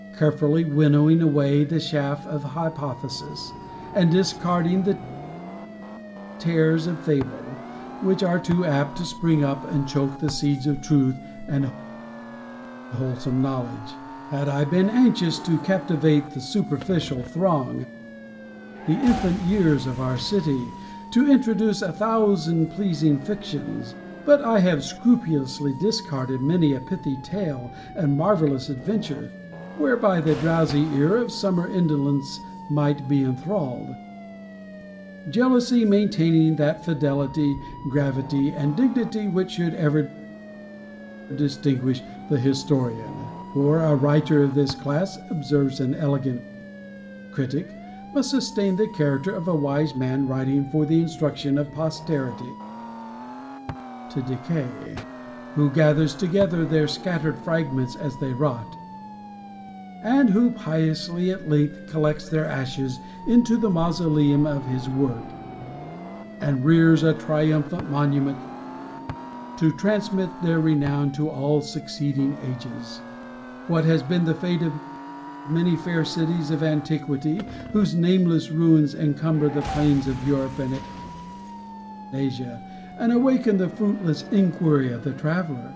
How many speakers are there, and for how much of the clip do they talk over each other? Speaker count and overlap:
1, no overlap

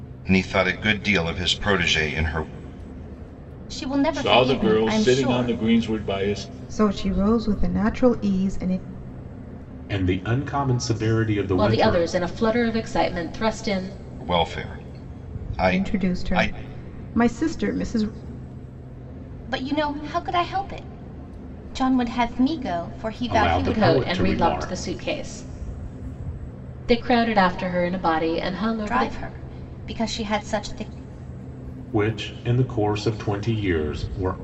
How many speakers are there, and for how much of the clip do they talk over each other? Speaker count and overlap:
6, about 14%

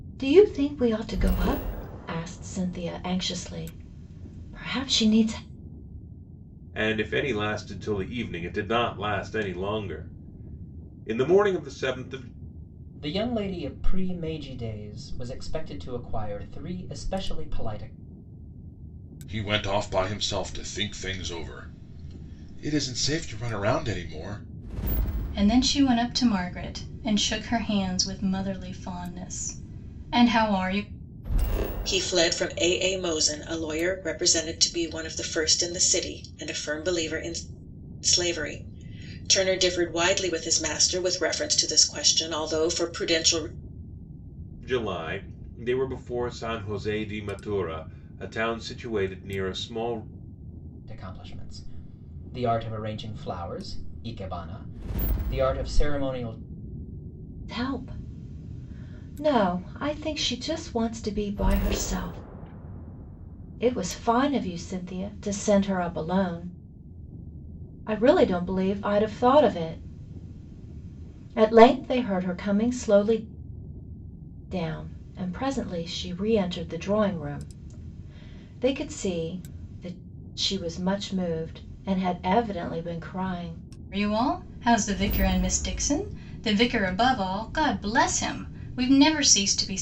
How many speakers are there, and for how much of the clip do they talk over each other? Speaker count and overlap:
6, no overlap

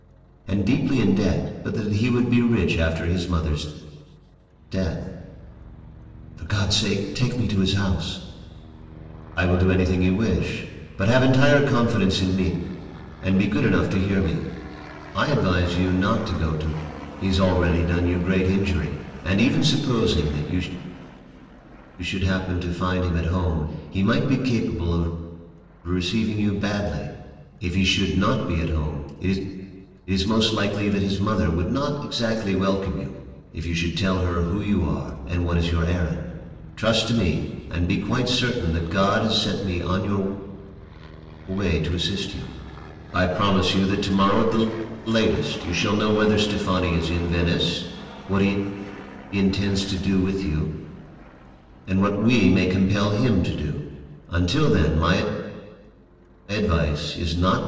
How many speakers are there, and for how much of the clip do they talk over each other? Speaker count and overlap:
1, no overlap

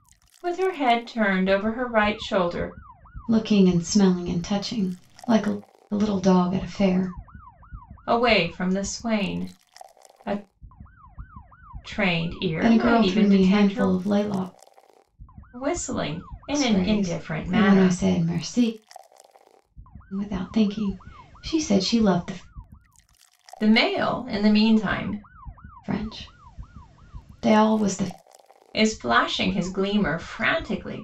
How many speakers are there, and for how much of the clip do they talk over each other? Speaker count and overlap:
2, about 9%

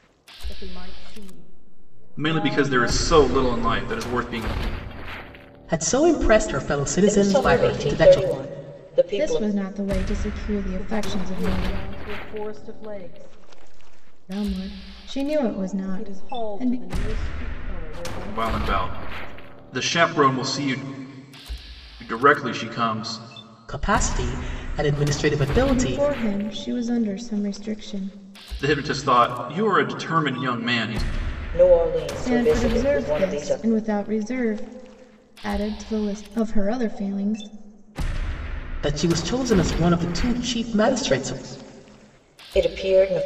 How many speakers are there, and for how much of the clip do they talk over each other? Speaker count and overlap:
5, about 17%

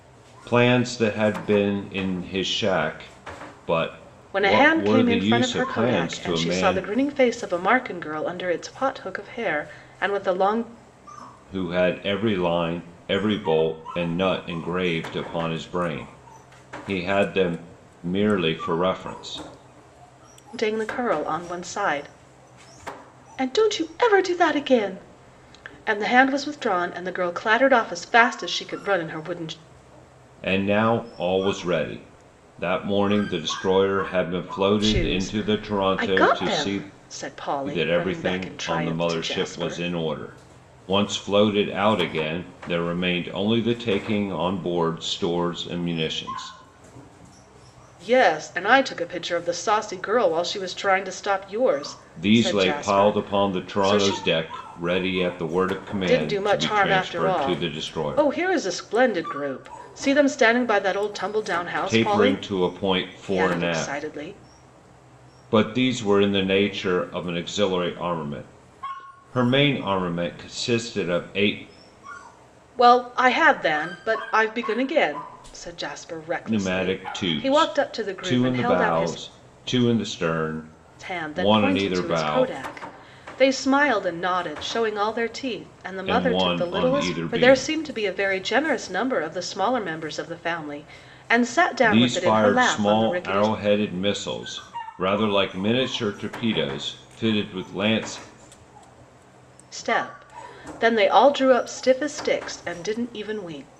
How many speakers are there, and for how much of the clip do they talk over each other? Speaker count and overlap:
2, about 20%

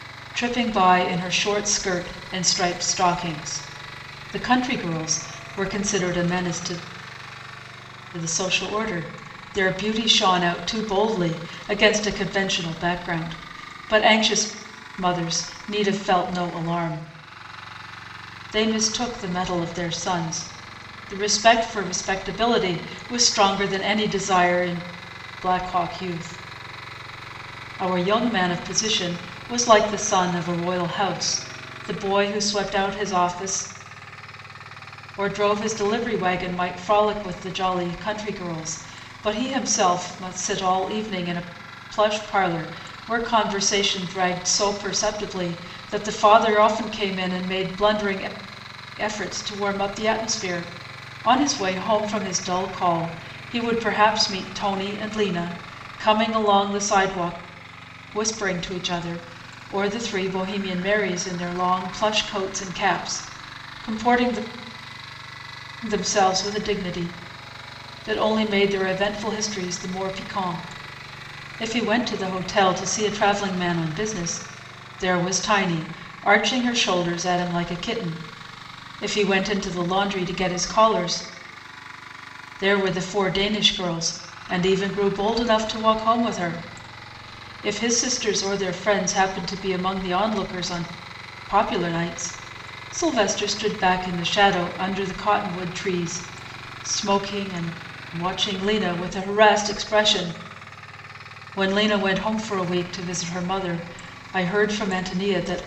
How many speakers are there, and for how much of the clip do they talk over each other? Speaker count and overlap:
1, no overlap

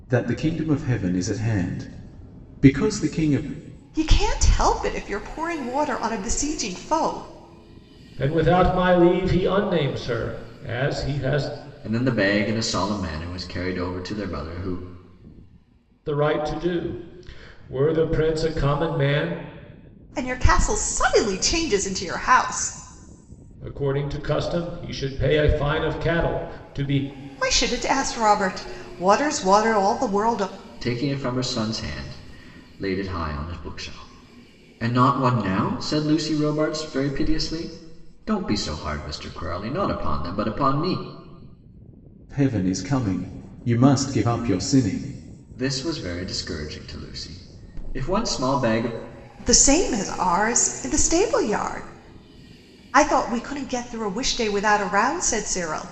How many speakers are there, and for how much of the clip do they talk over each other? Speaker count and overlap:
4, no overlap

